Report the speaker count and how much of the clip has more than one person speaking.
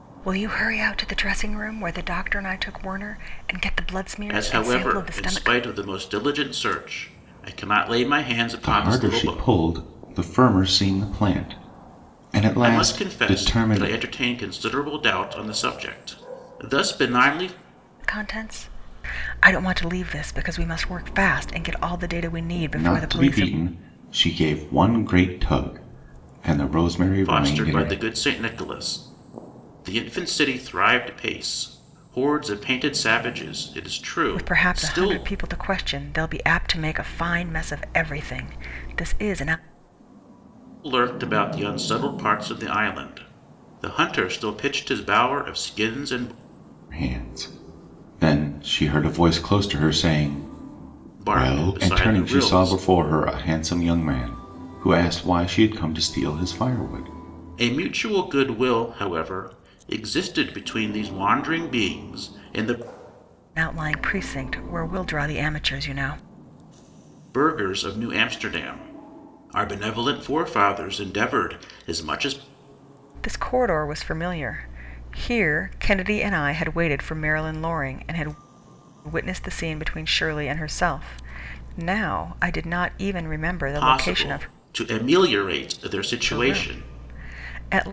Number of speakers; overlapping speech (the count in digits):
3, about 10%